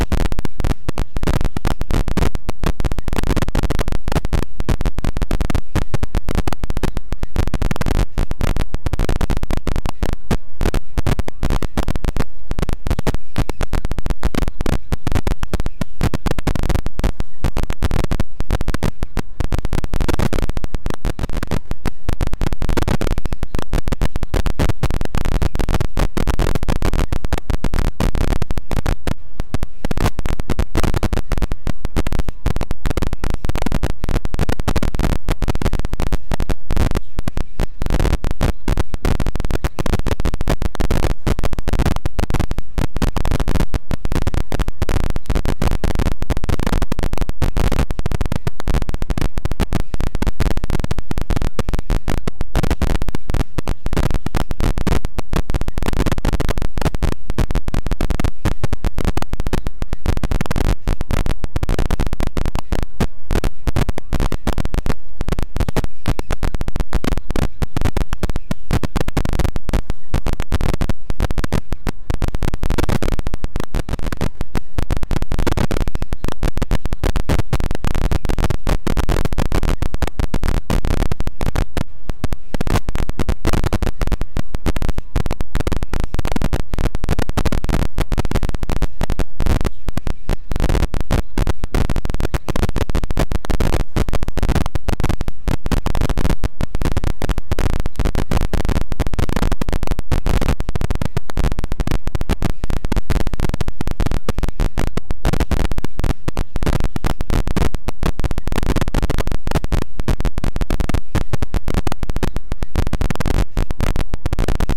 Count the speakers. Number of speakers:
0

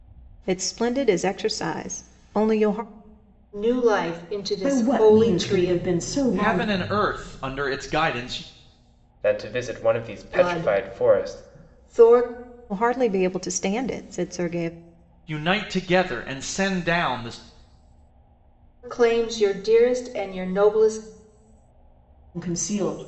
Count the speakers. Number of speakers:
5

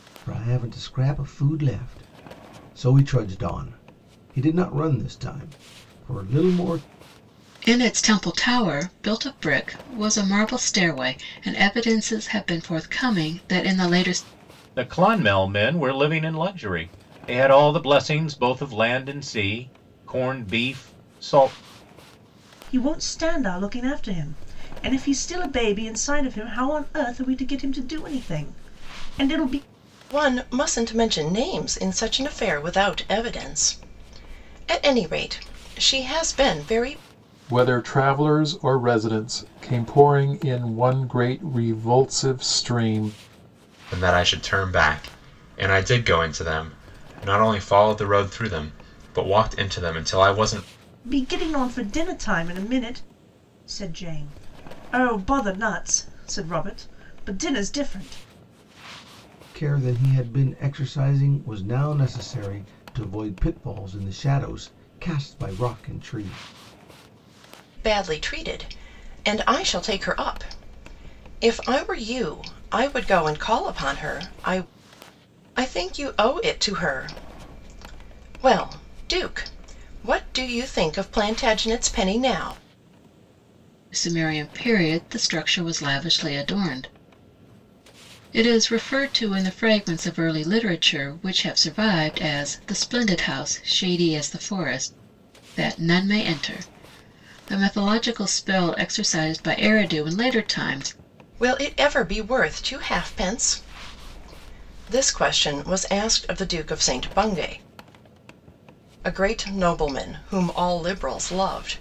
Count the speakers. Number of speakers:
7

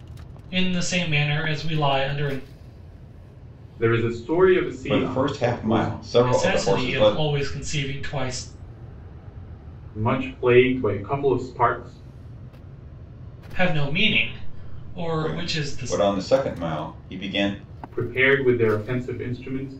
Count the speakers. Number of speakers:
3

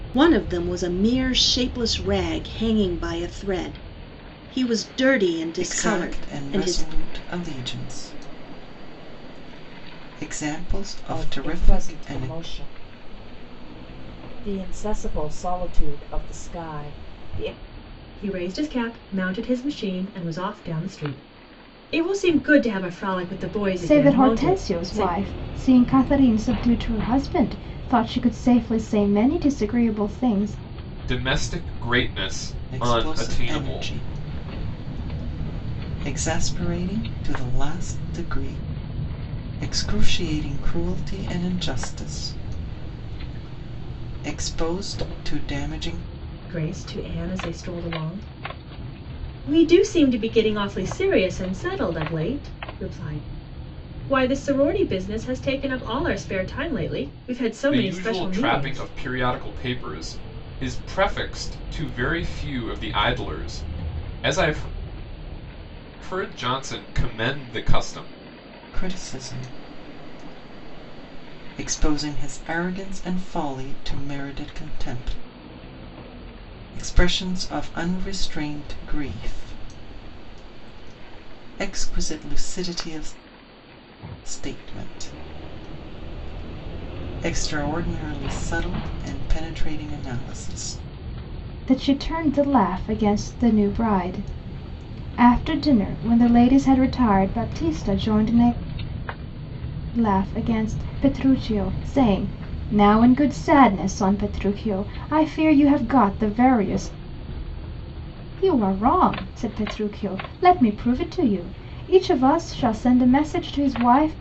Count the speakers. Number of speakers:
6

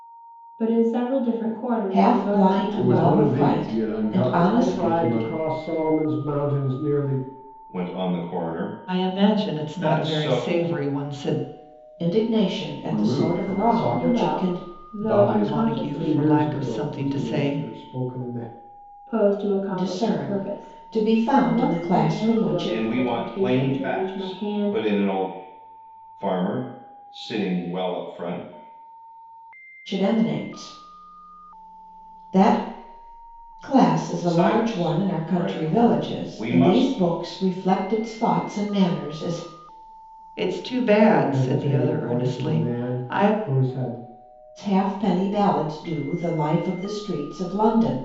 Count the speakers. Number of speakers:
6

